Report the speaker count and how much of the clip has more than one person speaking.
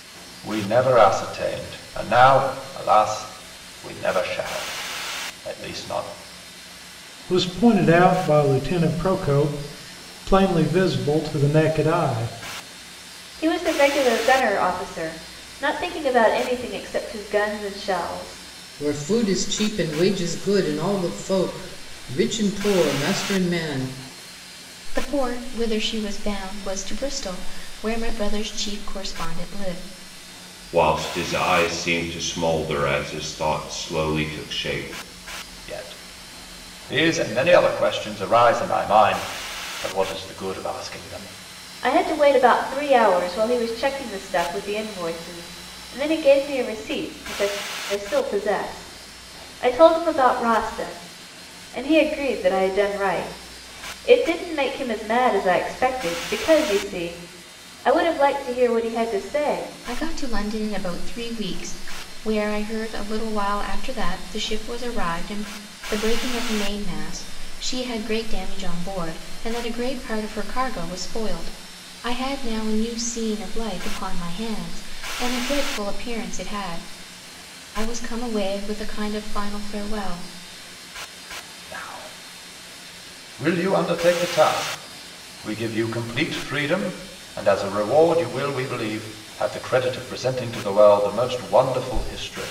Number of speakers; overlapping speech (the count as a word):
six, no overlap